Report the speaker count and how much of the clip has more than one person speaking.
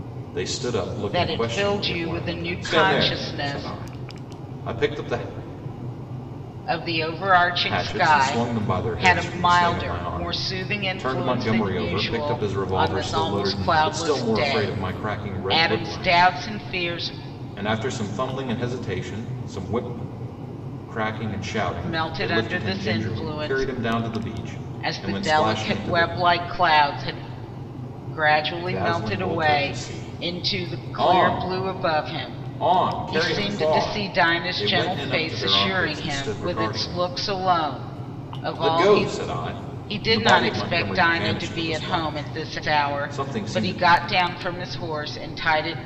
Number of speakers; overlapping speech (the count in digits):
2, about 56%